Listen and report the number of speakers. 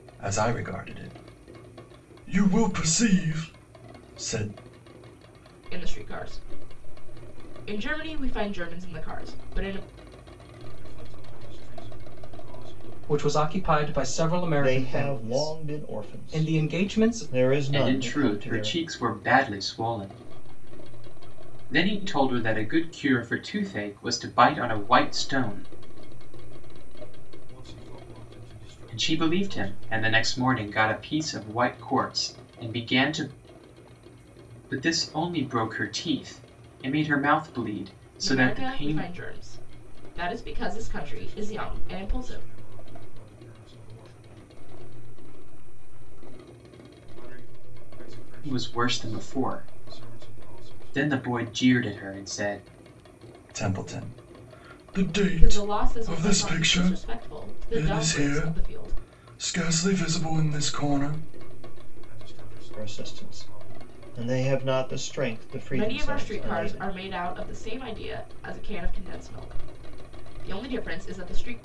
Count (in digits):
7